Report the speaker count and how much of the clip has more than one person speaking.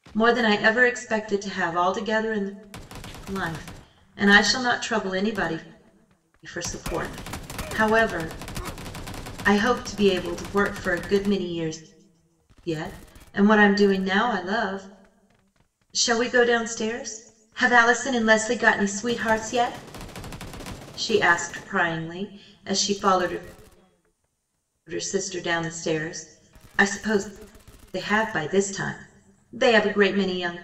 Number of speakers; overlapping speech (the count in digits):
1, no overlap